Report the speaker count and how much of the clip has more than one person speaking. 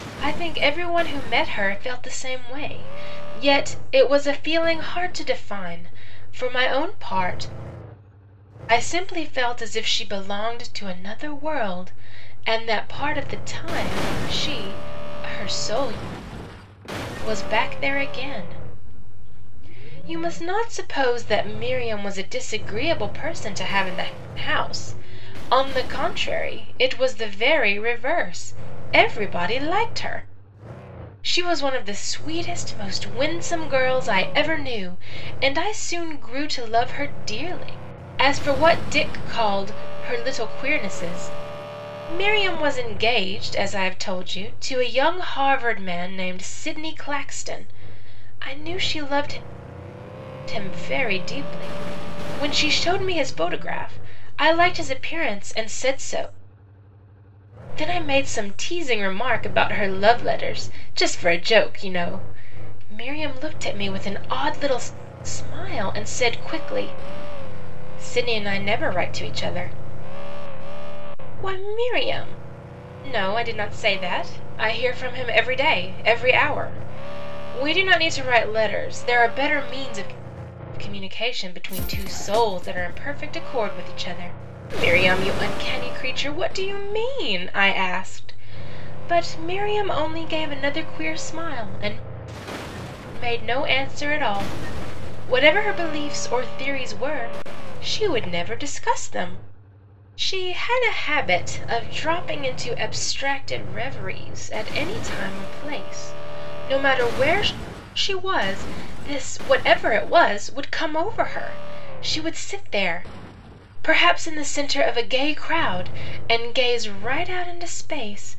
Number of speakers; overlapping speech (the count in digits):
1, no overlap